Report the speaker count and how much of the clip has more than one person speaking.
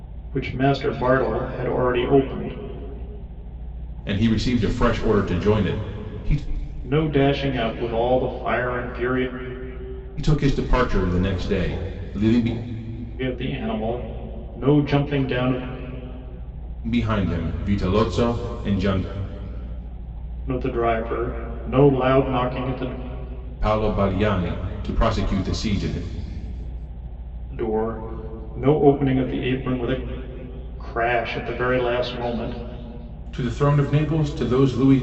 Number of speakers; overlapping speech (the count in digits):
2, no overlap